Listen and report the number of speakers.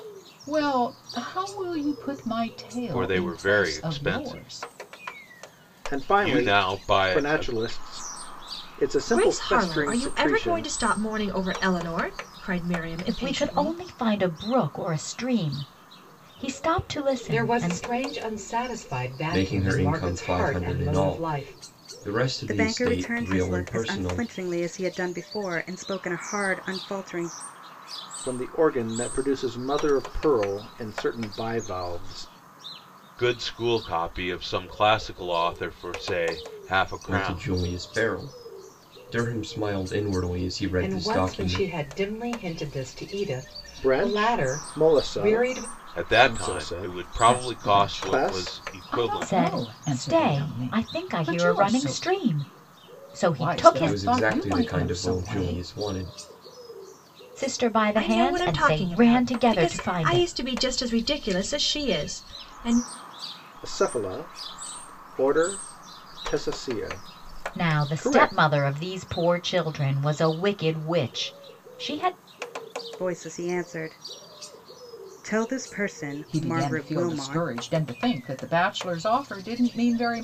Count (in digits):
8